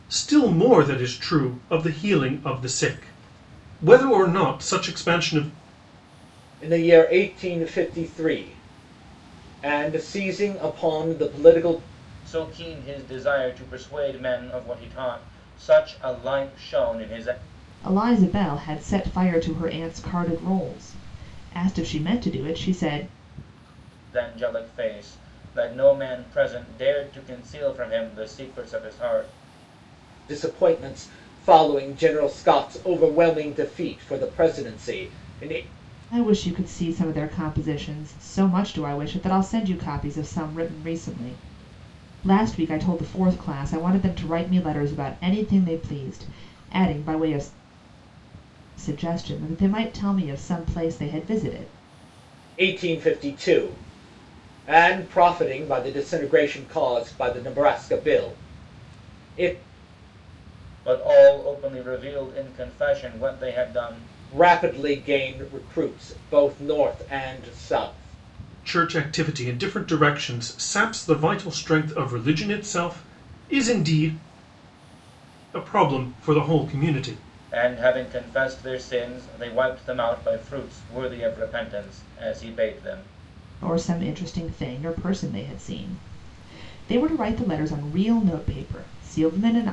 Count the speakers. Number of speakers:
4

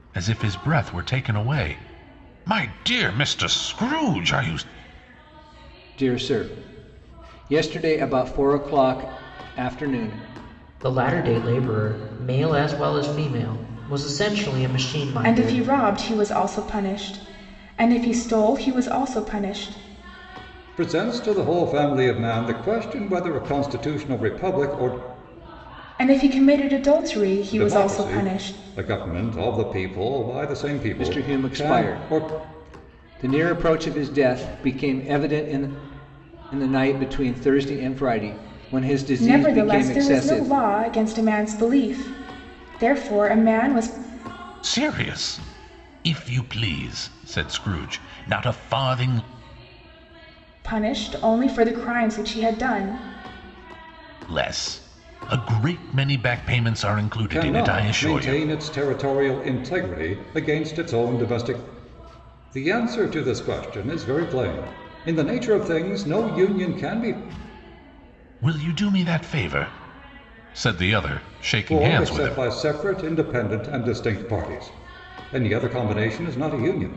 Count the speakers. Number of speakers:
5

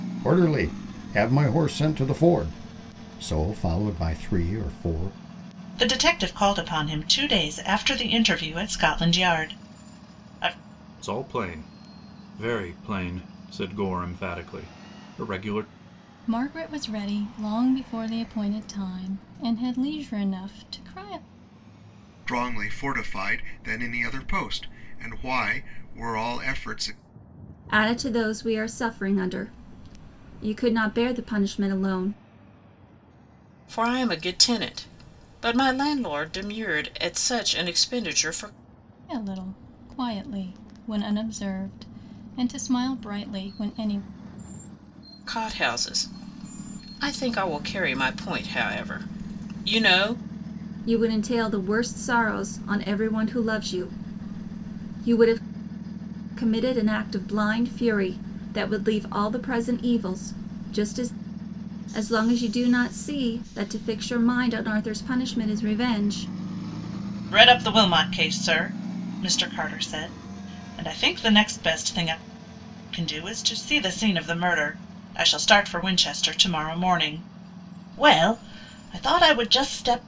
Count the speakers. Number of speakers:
7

